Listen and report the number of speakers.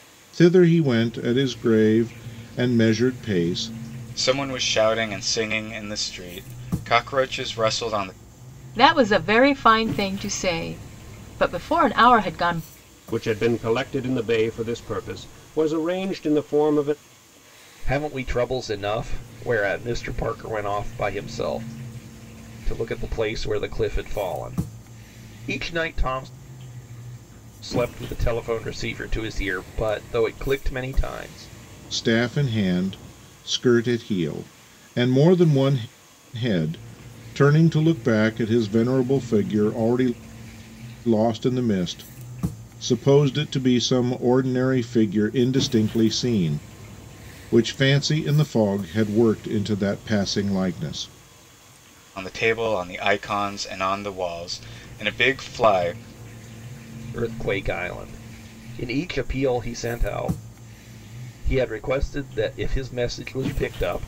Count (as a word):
five